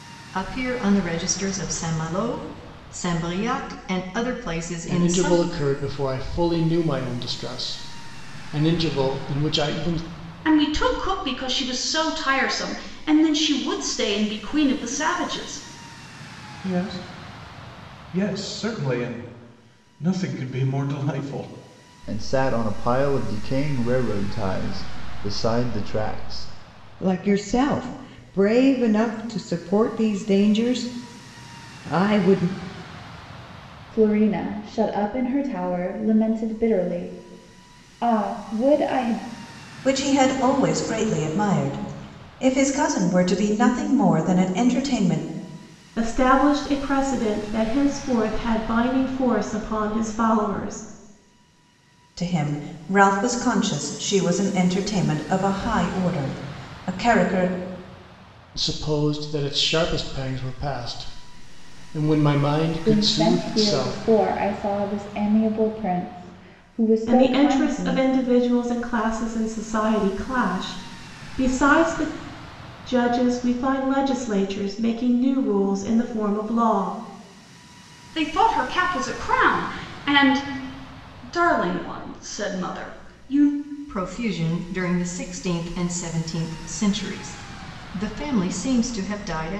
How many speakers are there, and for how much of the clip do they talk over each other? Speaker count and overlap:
nine, about 3%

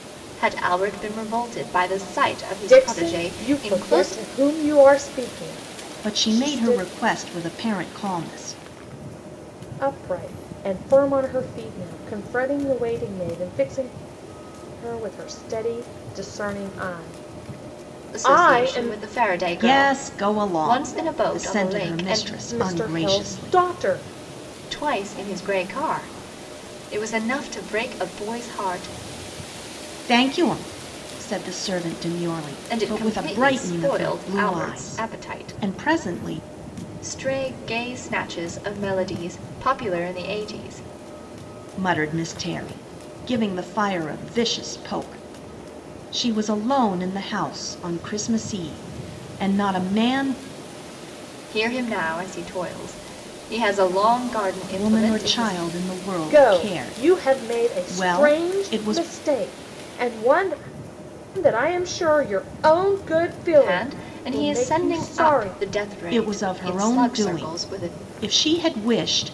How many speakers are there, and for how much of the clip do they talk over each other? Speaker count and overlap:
three, about 26%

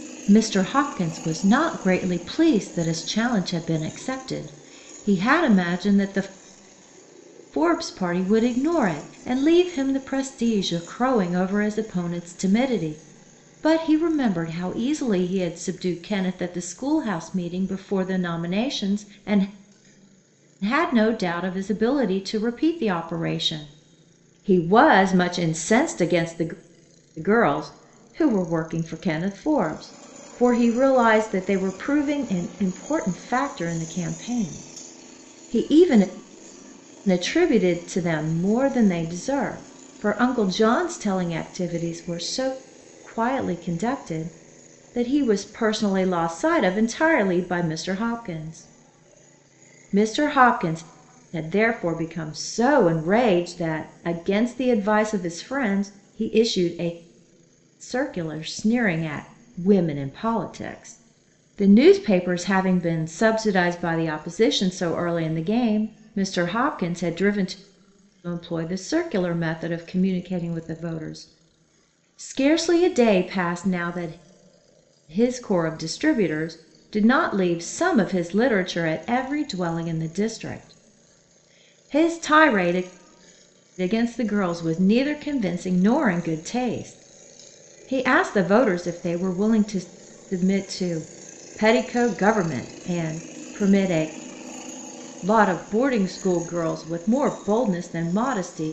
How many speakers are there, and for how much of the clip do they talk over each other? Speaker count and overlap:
one, no overlap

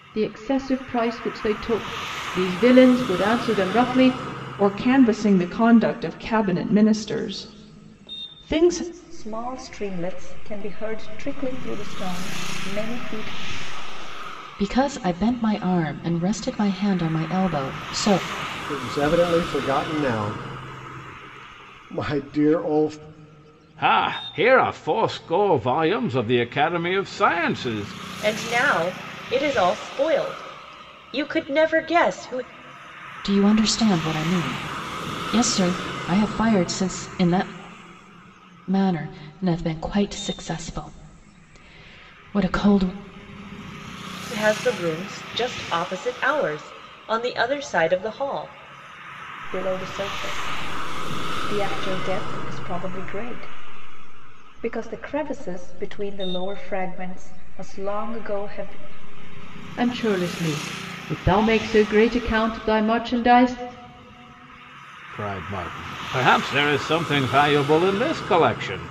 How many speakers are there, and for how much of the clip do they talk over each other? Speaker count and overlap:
seven, no overlap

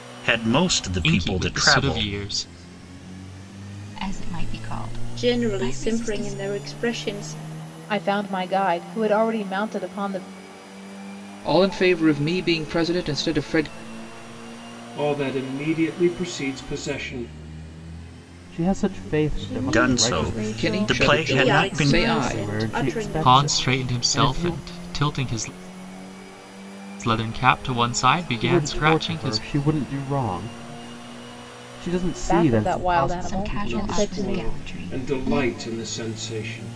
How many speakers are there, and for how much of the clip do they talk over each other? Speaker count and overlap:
nine, about 33%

